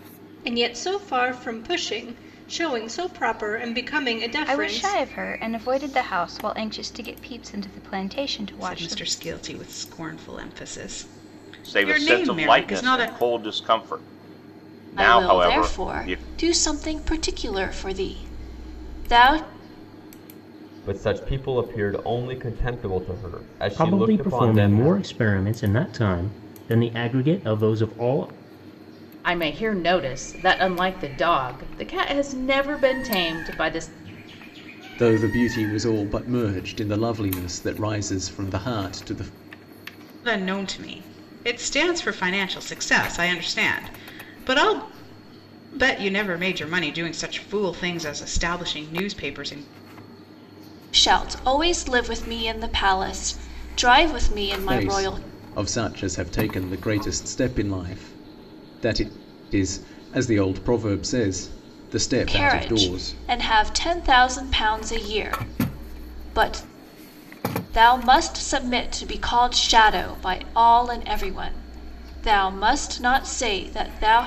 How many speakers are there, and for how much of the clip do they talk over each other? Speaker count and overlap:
9, about 9%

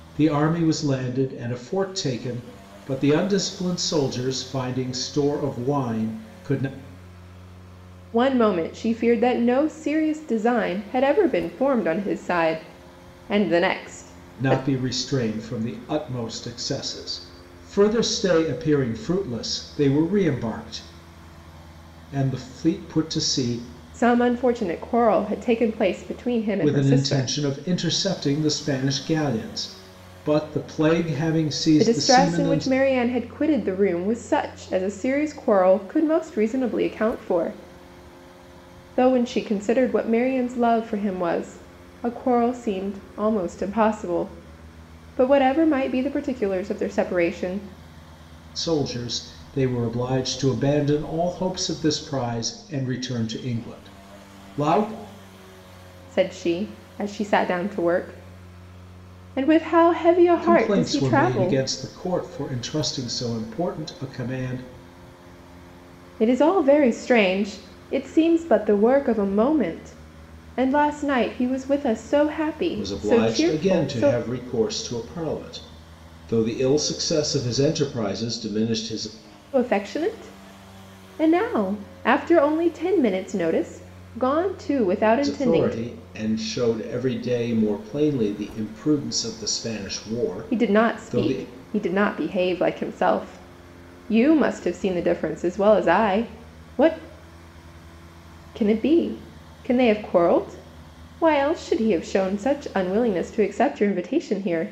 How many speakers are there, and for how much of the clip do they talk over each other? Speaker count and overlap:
2, about 6%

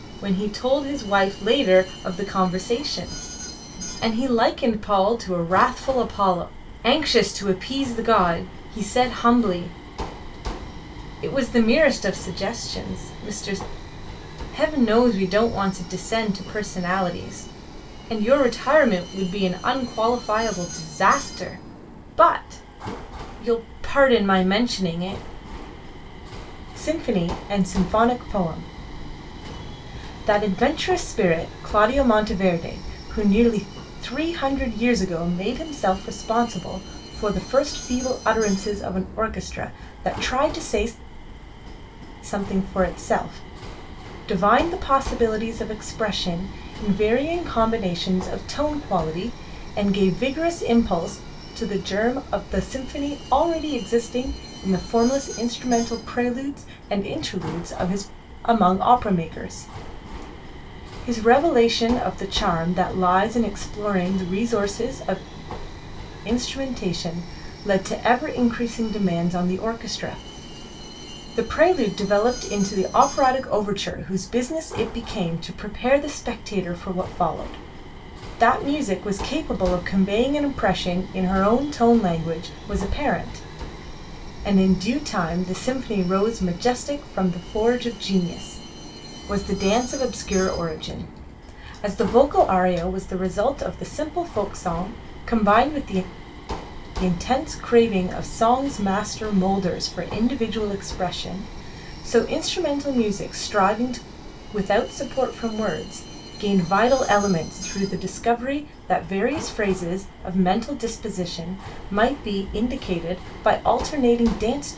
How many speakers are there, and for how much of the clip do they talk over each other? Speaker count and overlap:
1, no overlap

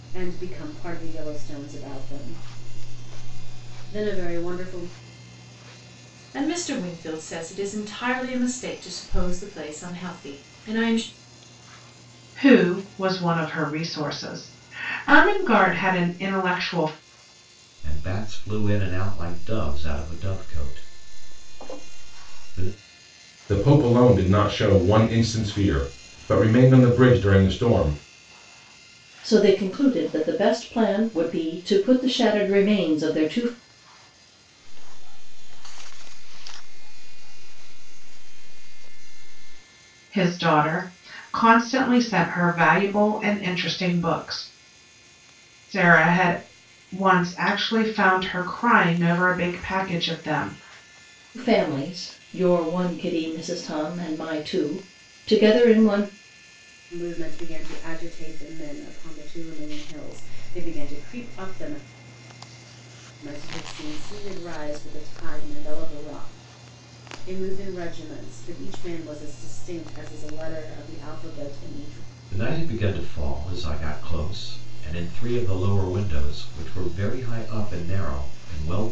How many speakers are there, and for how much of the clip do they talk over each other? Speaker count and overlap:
7, no overlap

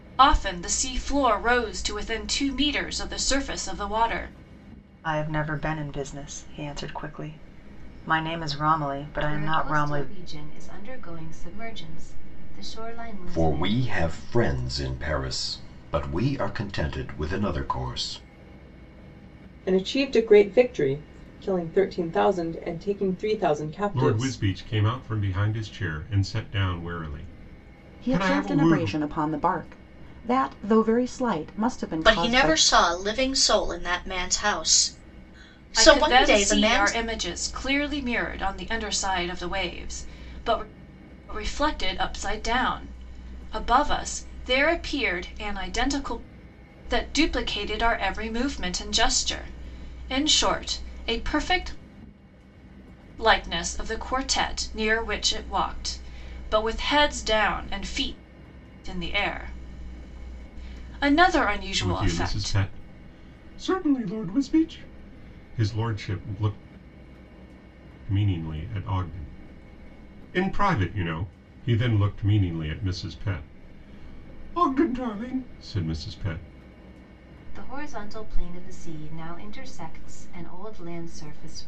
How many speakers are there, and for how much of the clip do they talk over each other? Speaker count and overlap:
8, about 7%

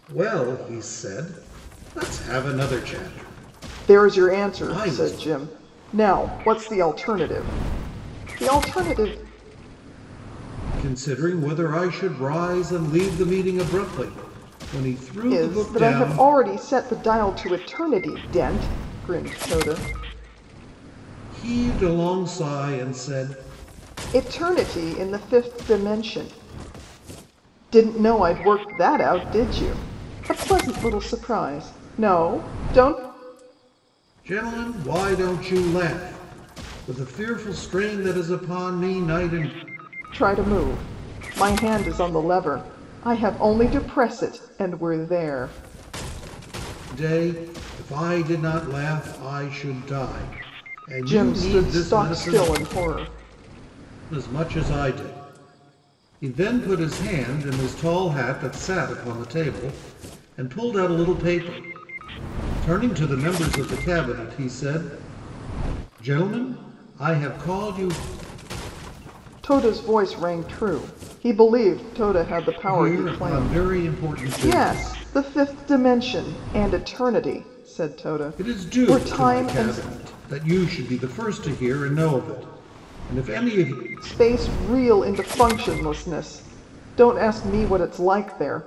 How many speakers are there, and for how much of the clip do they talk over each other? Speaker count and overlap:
2, about 8%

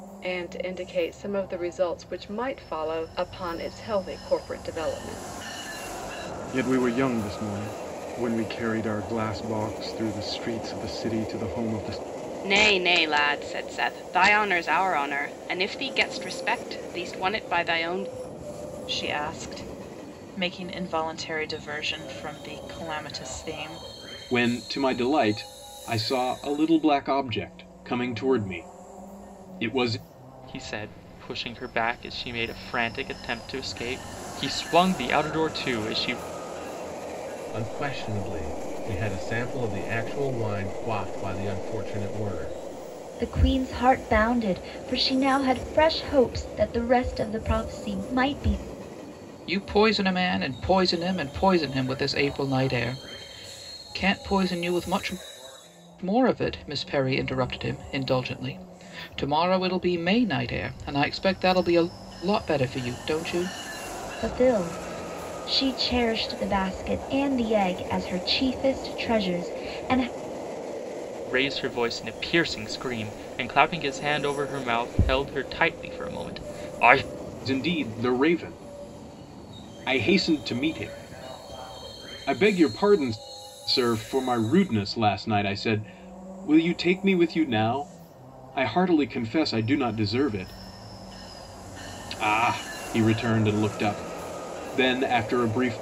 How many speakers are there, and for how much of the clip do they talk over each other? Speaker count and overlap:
9, no overlap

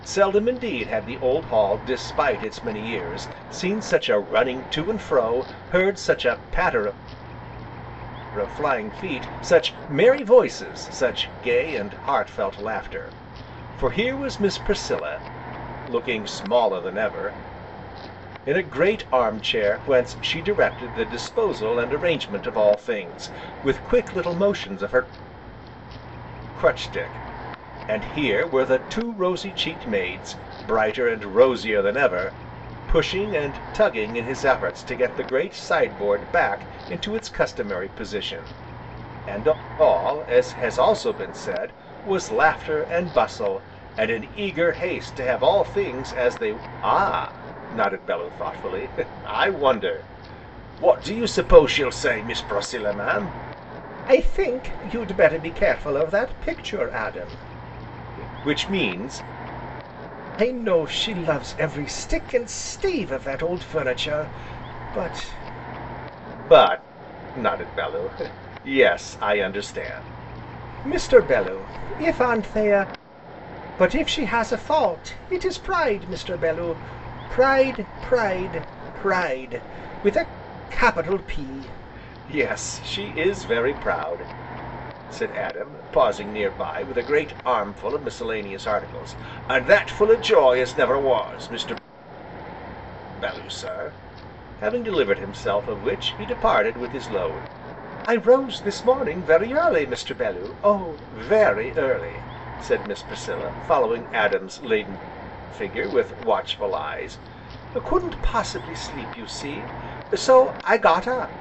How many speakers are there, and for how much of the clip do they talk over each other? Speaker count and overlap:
1, no overlap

